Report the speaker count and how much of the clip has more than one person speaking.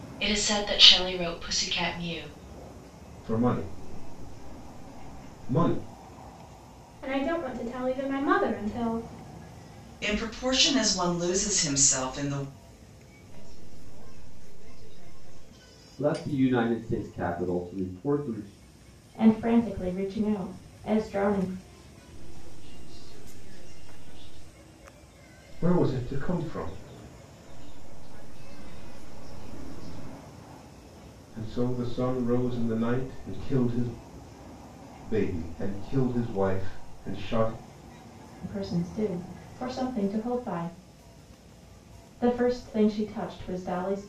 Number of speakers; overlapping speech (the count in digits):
7, no overlap